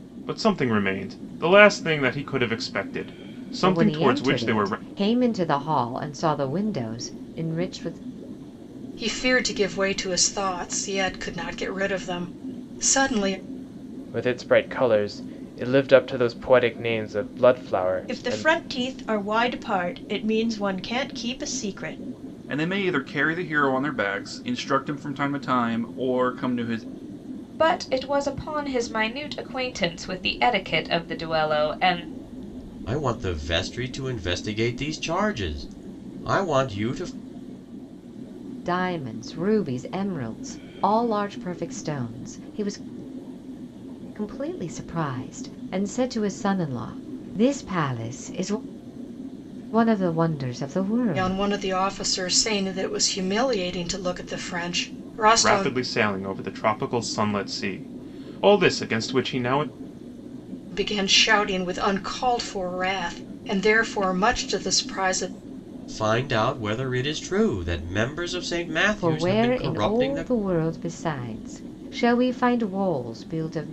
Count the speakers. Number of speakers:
8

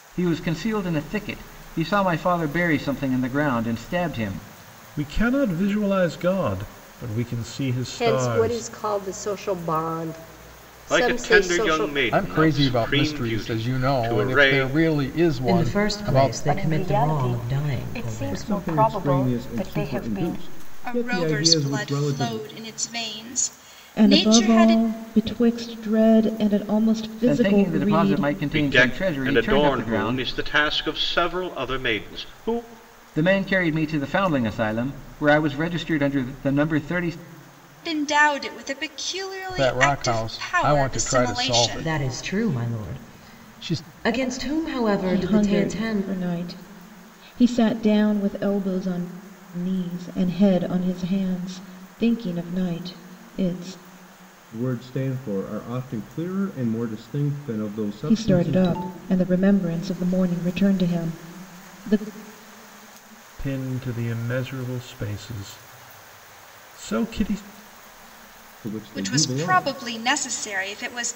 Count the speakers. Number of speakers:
10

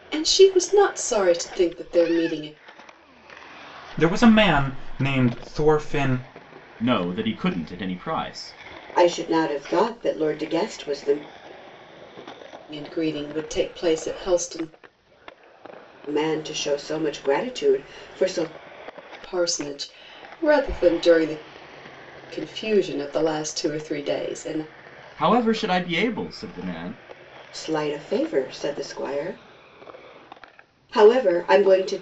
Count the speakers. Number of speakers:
4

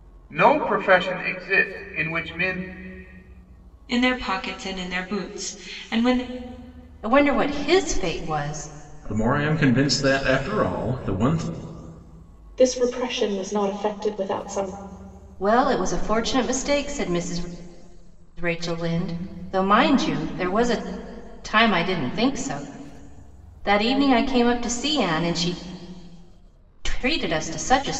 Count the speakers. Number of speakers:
5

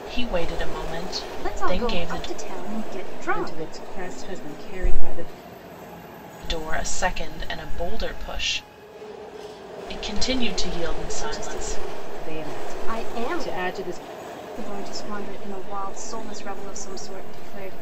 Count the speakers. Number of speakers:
3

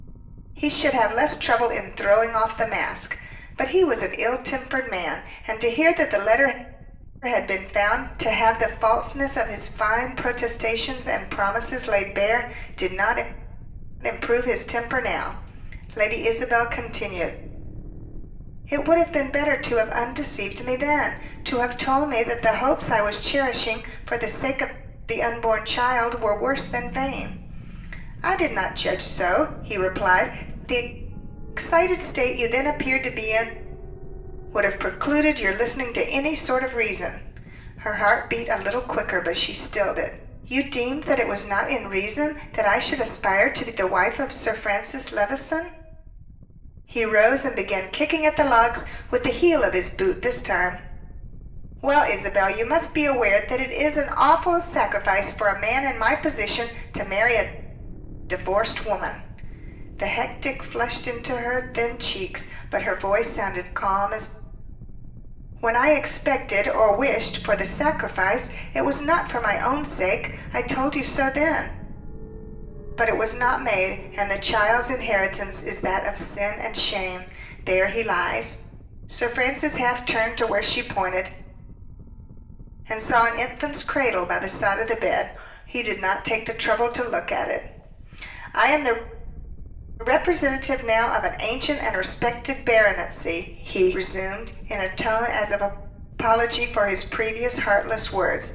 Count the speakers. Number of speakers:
1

